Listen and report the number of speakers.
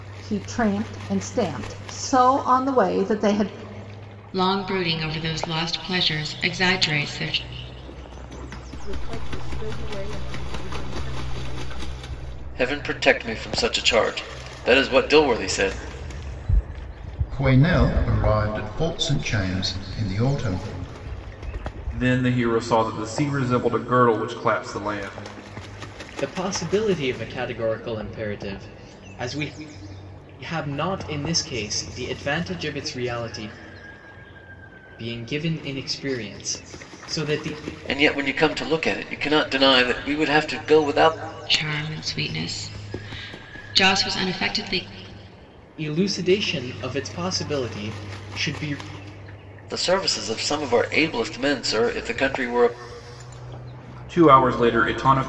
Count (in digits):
7